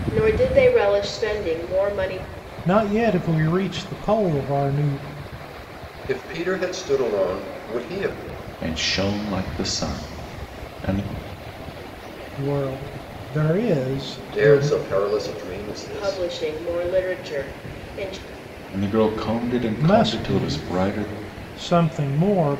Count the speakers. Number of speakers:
4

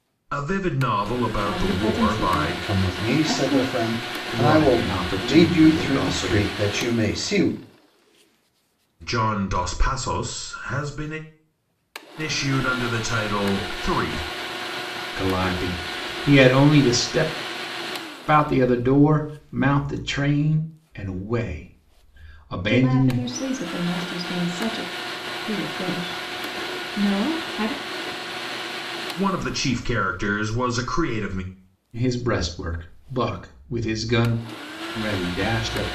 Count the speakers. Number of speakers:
4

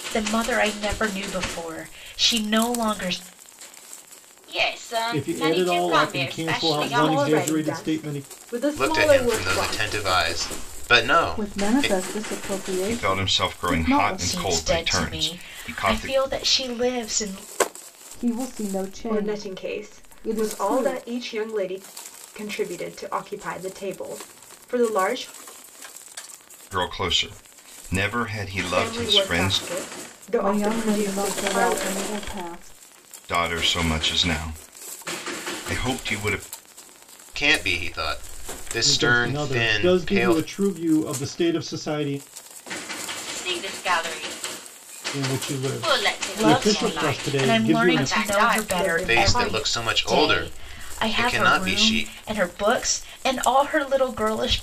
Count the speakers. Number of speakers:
7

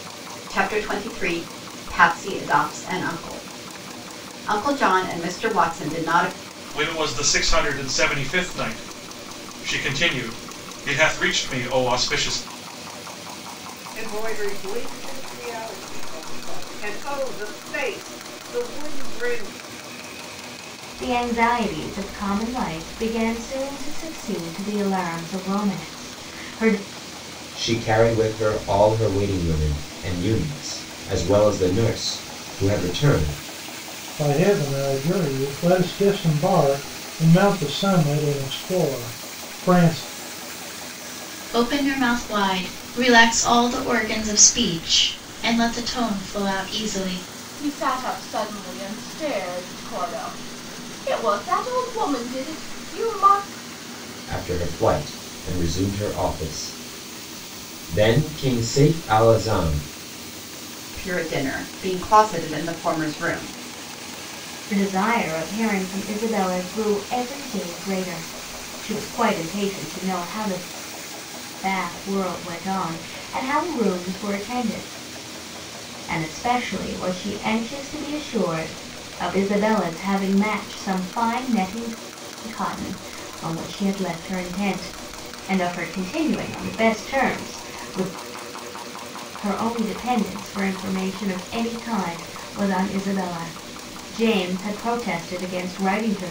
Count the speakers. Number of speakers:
8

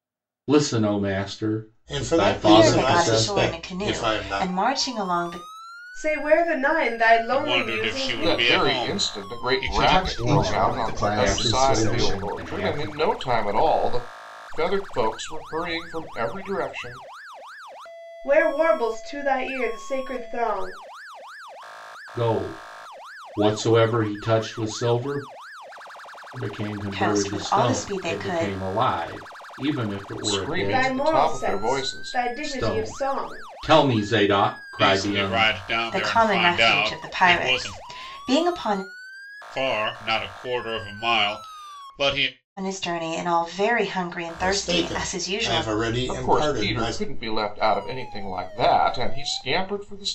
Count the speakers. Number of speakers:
7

